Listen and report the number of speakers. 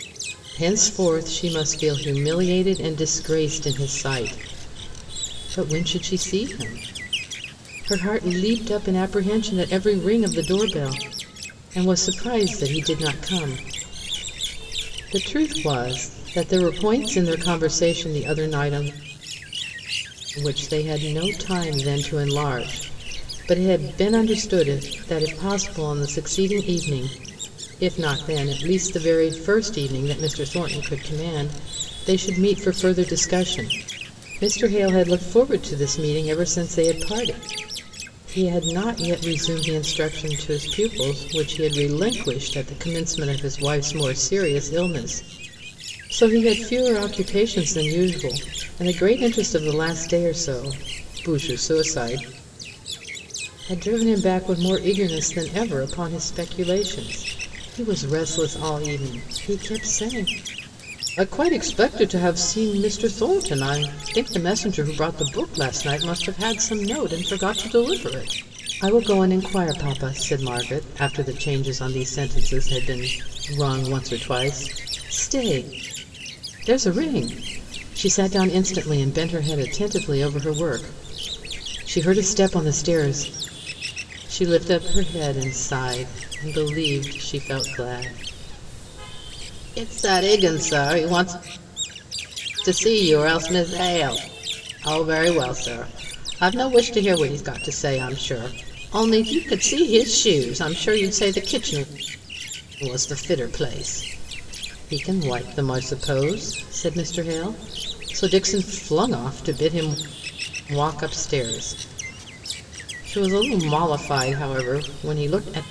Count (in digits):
1